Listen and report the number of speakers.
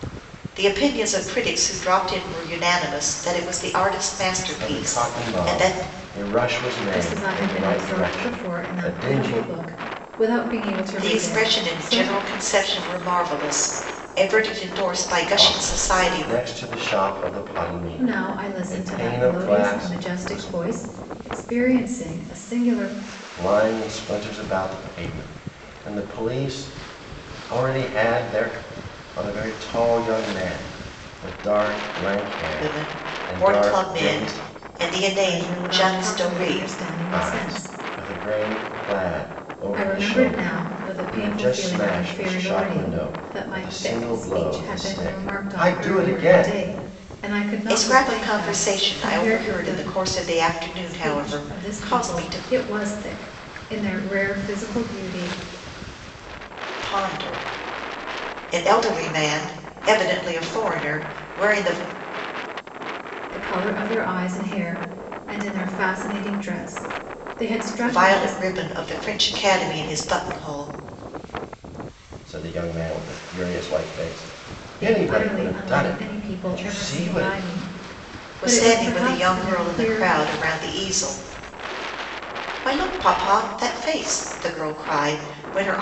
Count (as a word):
three